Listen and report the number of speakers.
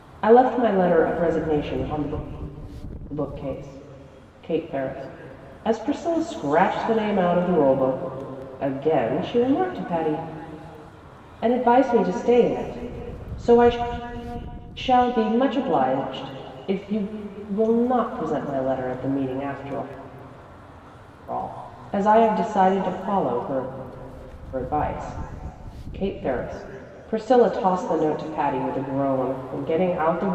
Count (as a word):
one